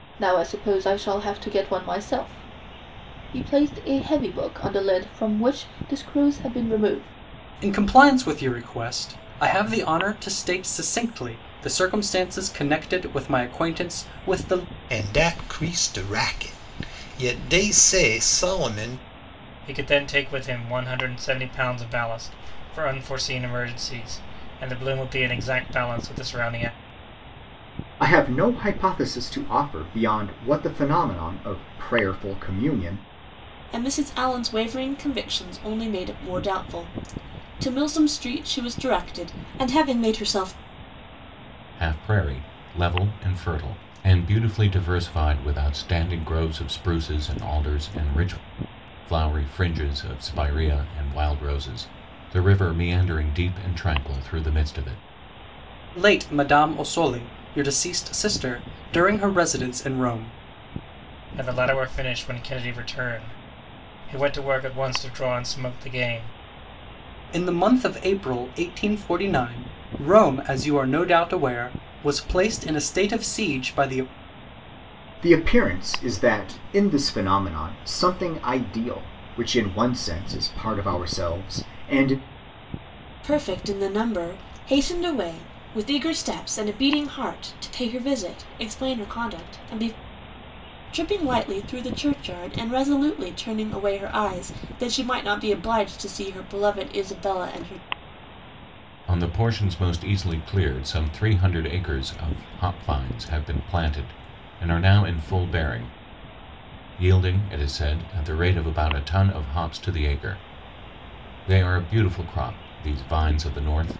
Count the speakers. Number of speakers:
seven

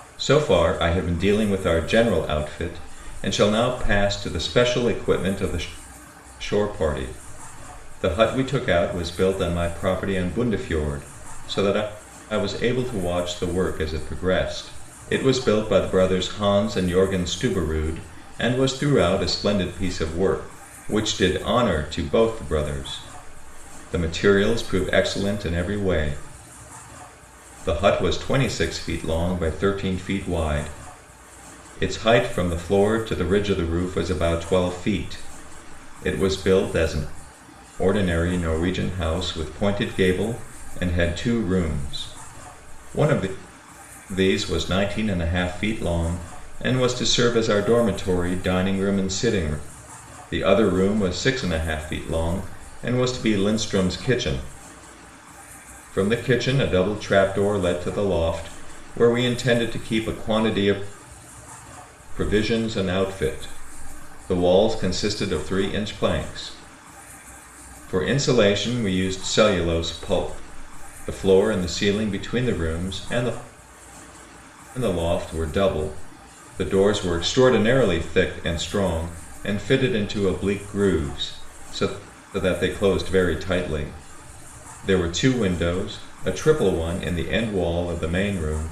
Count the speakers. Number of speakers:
one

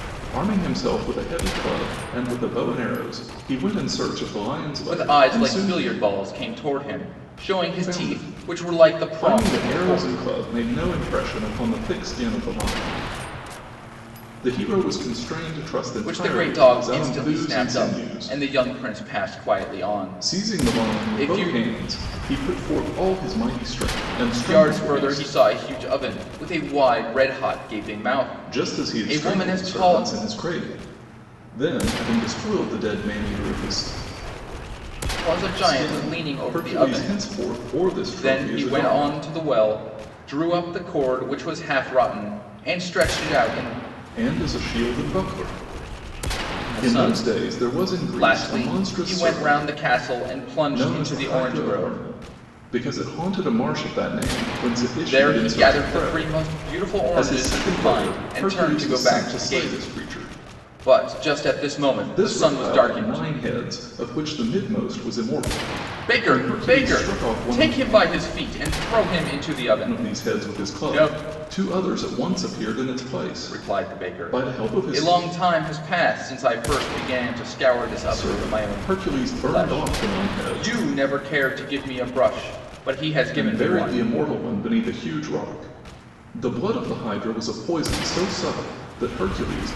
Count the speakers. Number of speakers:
two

